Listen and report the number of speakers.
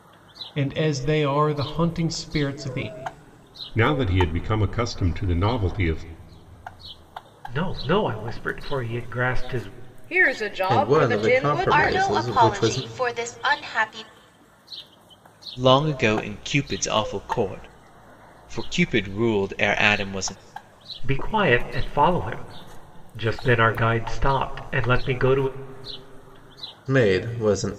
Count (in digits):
7